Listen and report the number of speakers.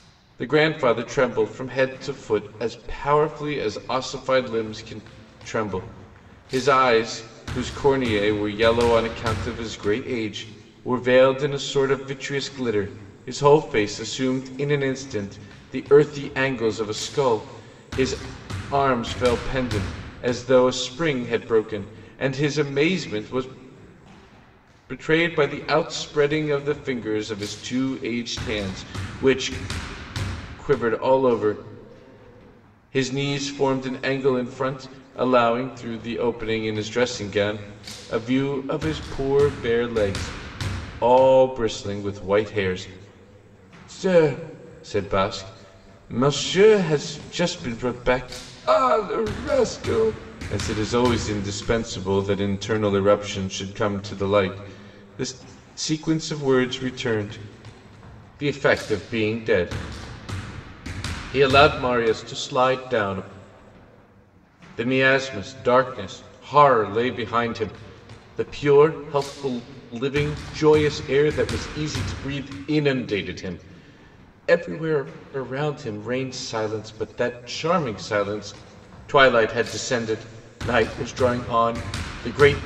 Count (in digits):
1